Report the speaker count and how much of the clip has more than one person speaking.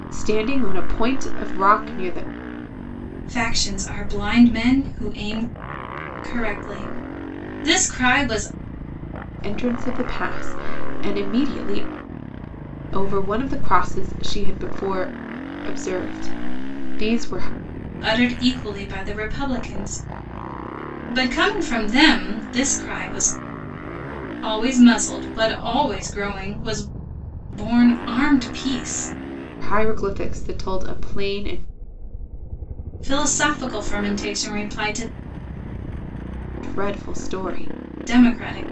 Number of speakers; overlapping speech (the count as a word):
two, no overlap